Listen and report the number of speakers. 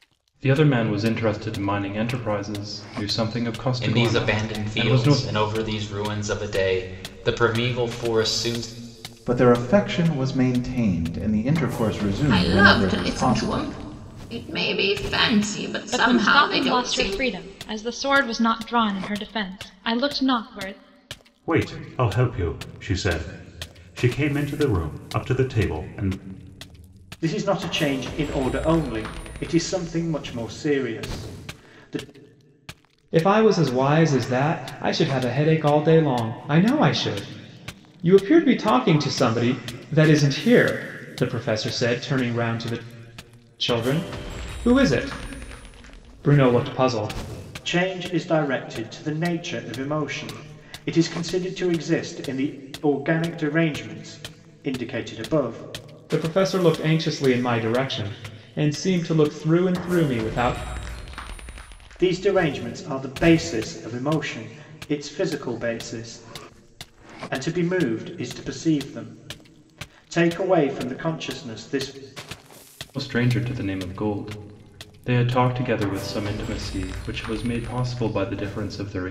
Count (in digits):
8